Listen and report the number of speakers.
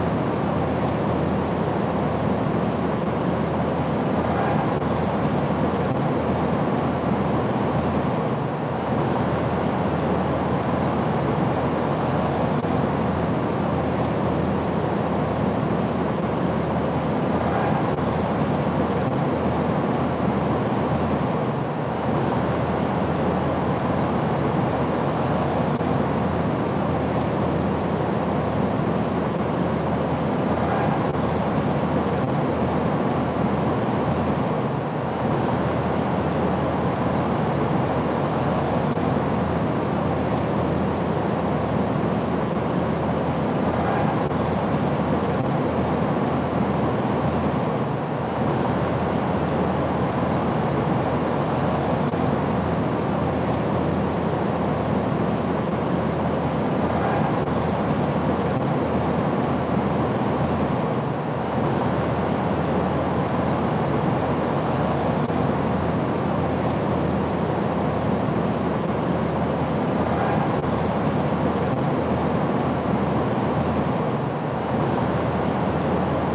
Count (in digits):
0